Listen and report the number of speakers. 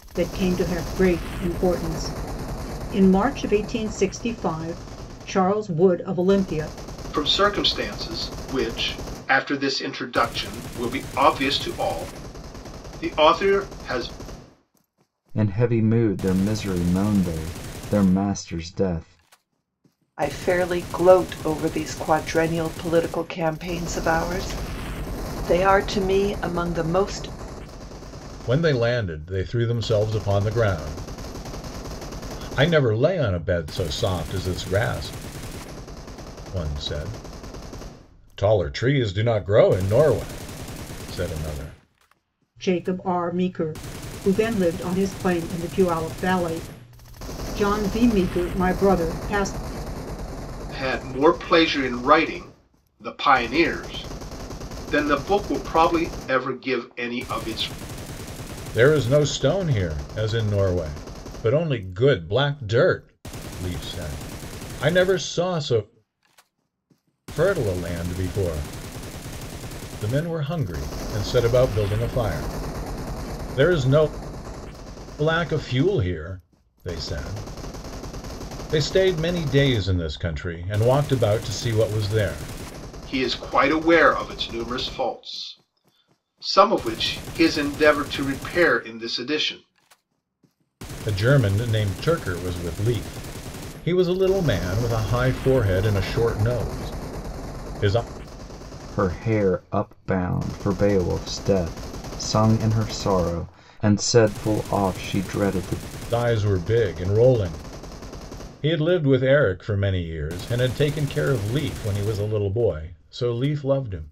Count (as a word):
five